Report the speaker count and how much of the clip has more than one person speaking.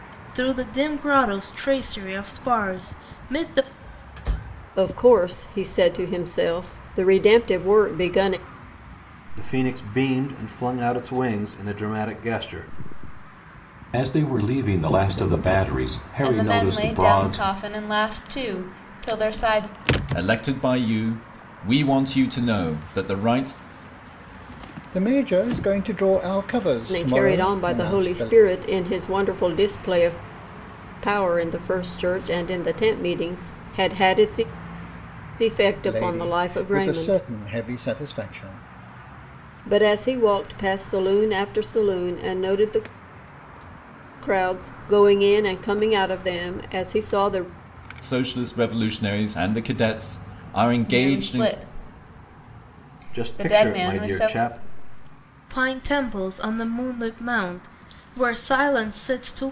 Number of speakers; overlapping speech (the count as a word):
seven, about 10%